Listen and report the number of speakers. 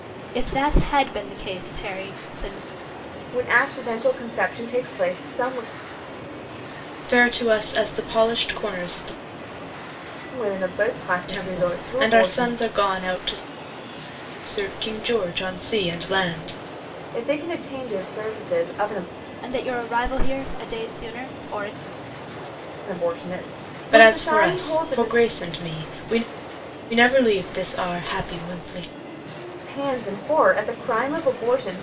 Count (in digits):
3